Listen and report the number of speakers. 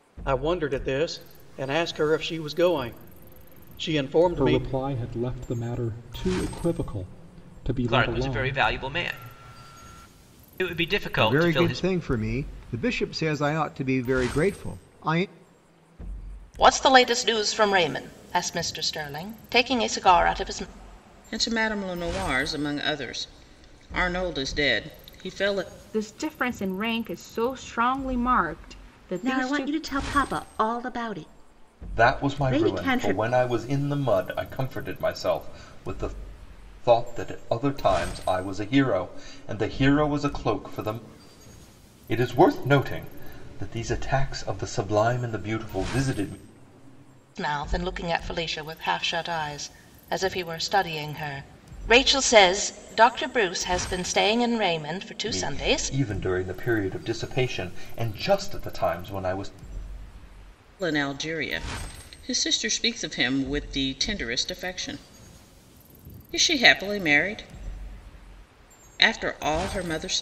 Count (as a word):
nine